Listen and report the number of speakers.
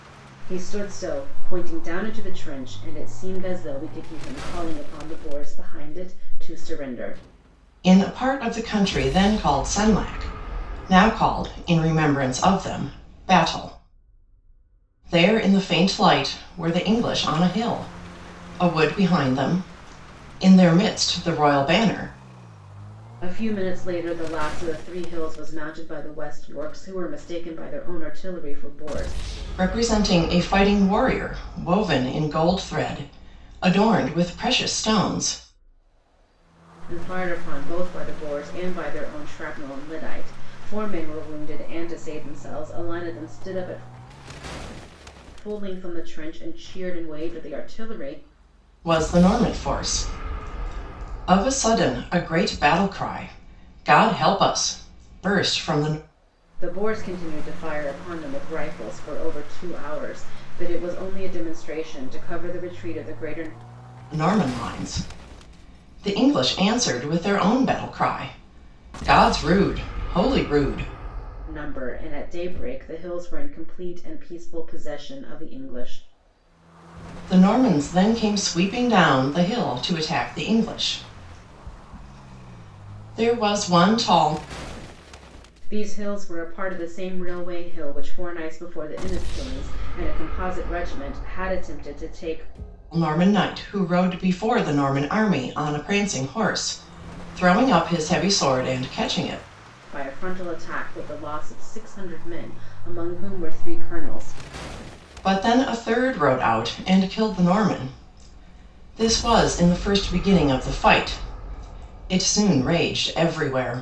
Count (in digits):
2